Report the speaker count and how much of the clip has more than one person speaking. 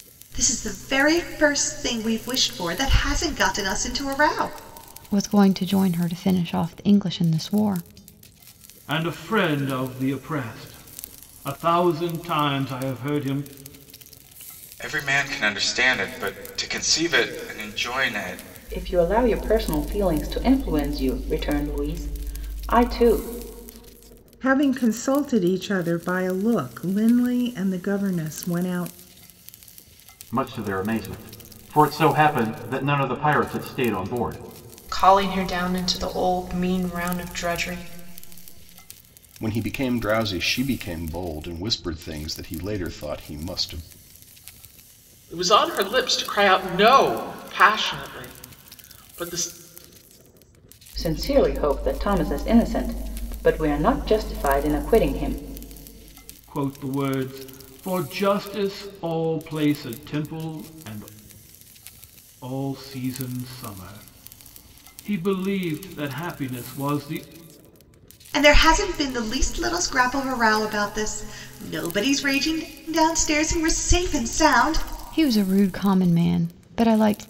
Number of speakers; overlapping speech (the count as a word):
ten, no overlap